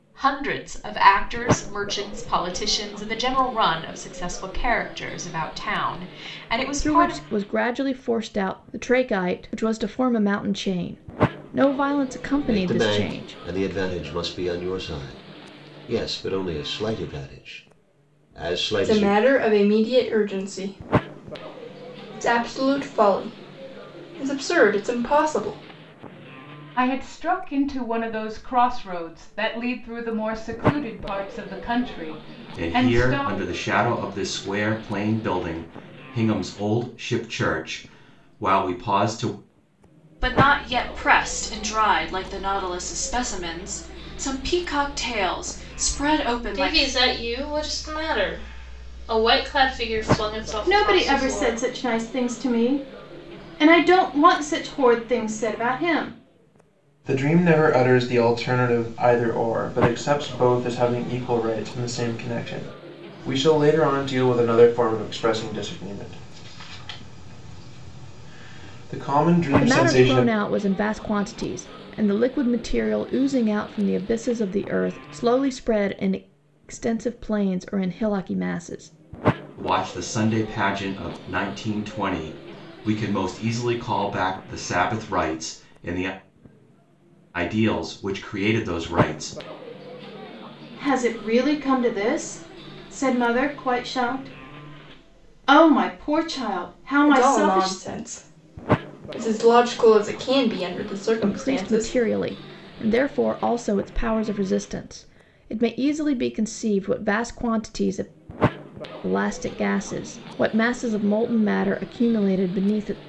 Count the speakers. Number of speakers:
10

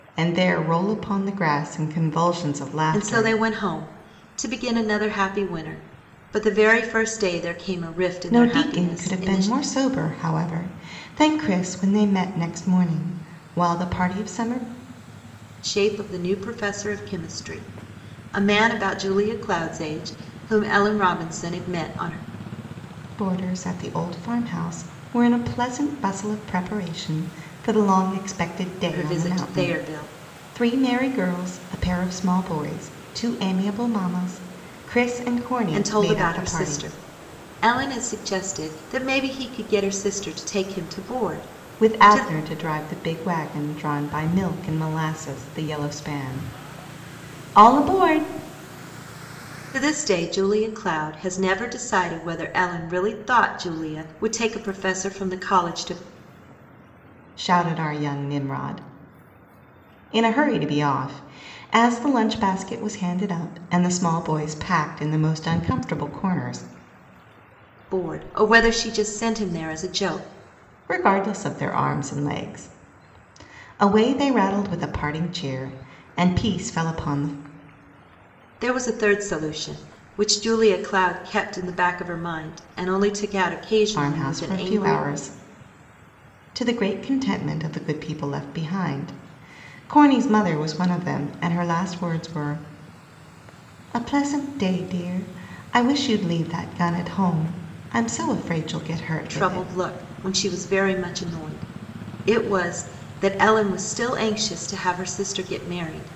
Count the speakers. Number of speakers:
2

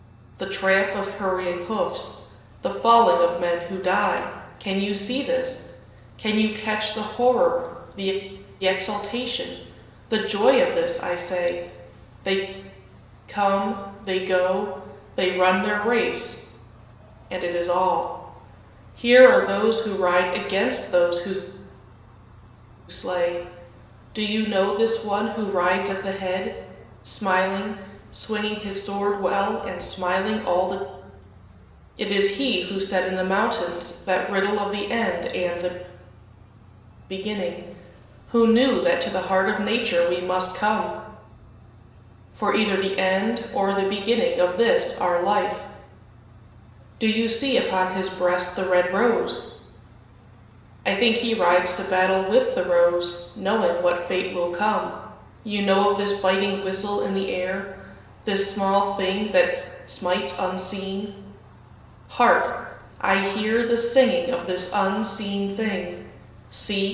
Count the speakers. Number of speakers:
1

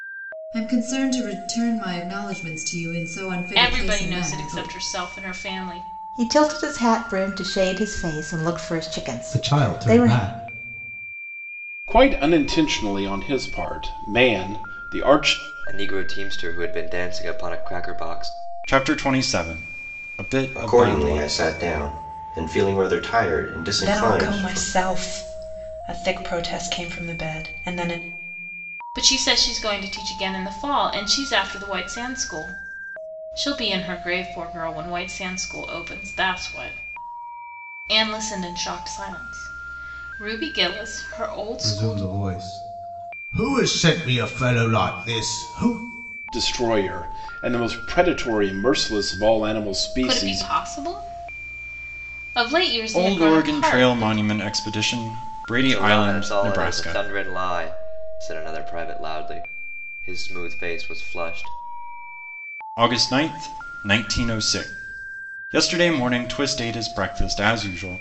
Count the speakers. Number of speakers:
9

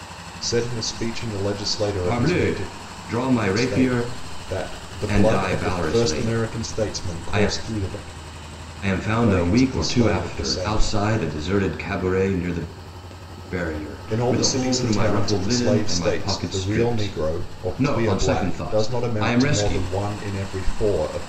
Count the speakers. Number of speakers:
2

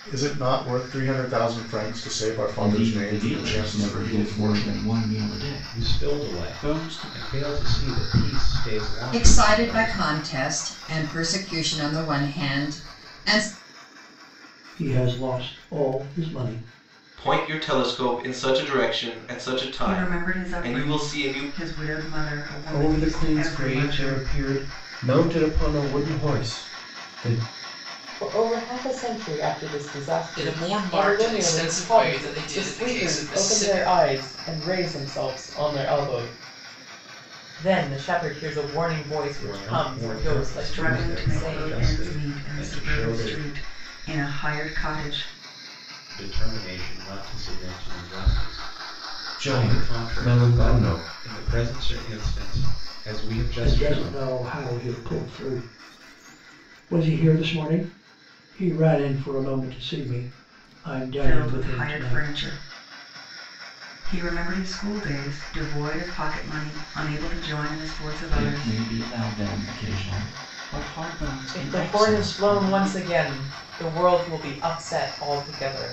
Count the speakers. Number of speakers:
10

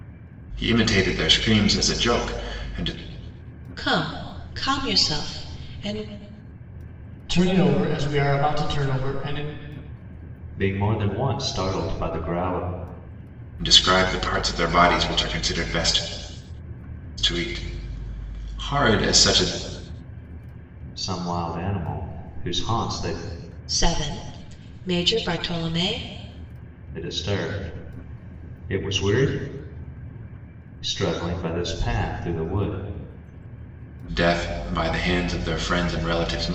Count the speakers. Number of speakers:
4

